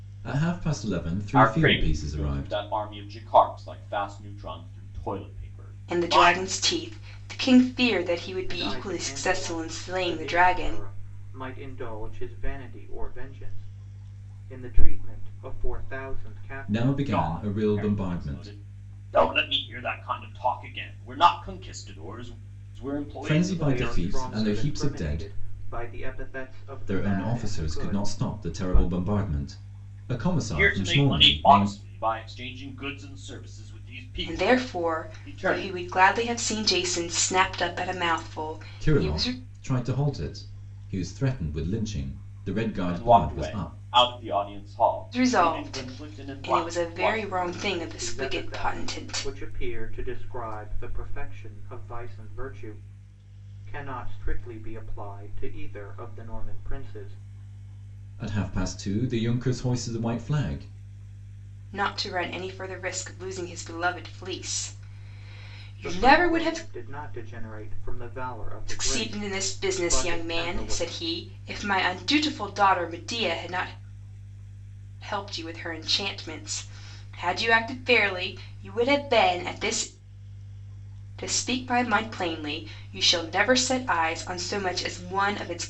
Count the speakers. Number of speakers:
four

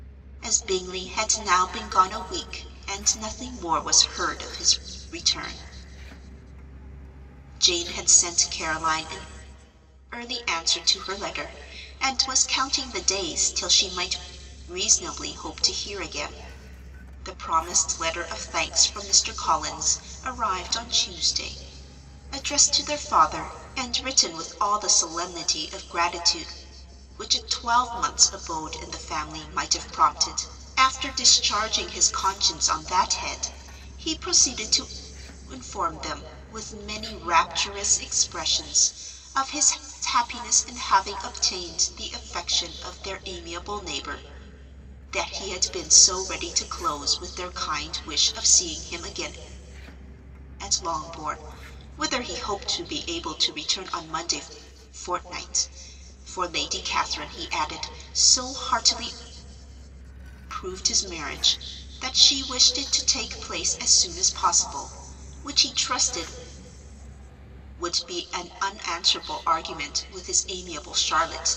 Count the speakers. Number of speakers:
one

